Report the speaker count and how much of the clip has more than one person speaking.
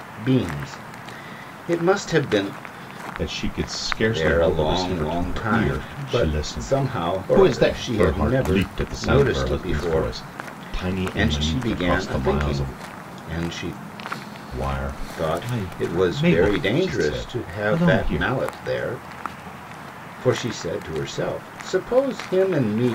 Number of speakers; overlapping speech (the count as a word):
two, about 48%